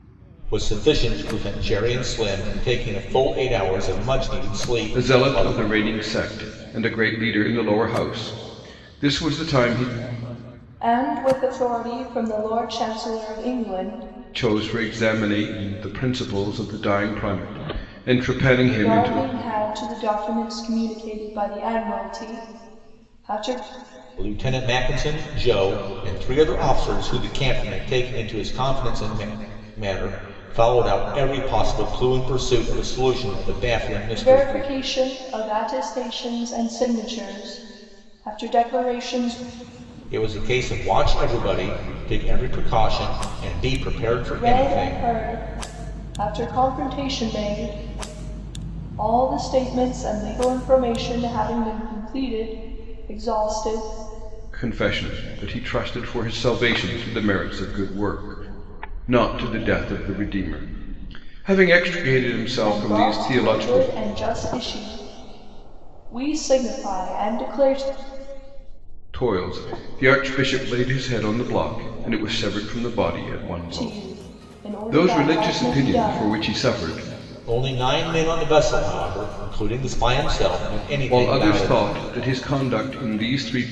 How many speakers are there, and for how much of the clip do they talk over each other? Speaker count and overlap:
three, about 8%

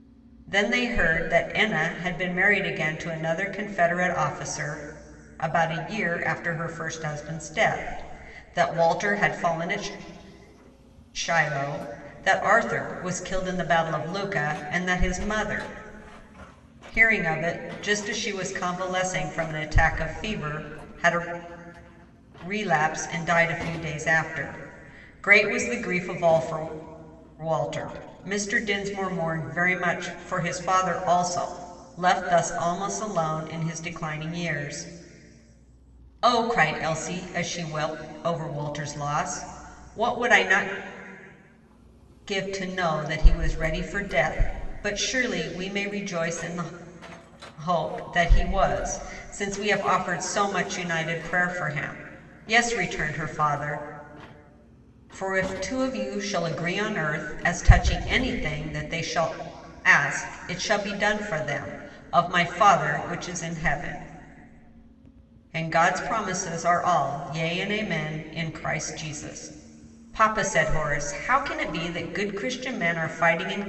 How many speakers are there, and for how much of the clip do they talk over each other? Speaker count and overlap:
one, no overlap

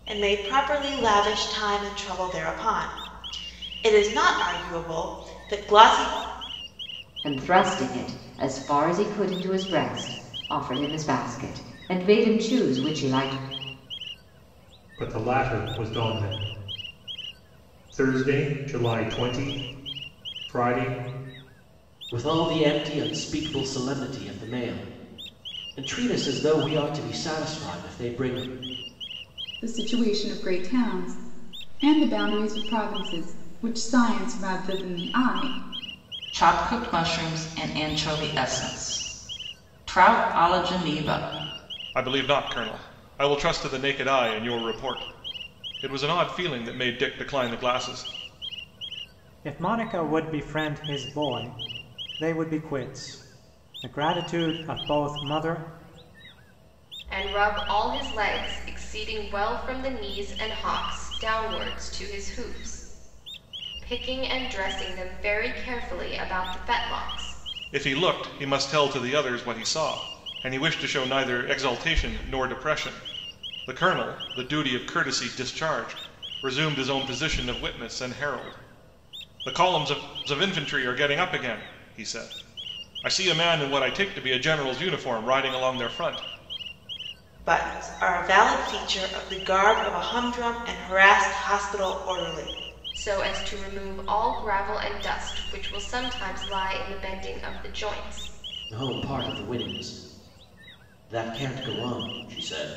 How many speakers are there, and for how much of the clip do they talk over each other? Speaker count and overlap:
nine, no overlap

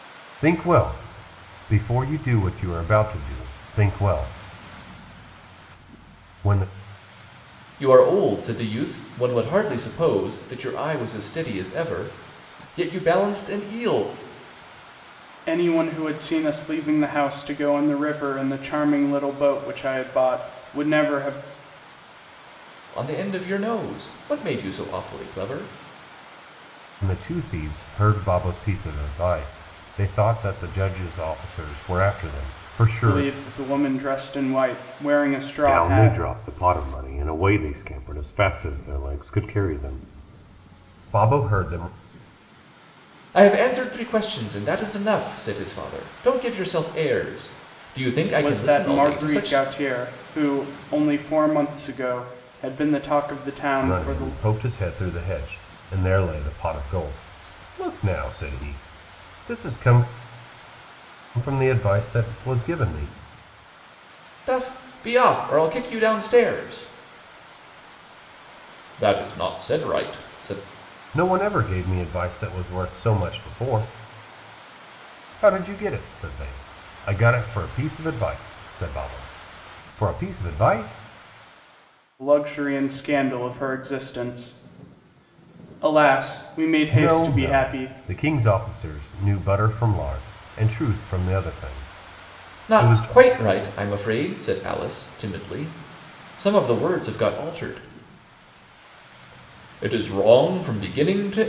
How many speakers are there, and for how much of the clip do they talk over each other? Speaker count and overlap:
three, about 4%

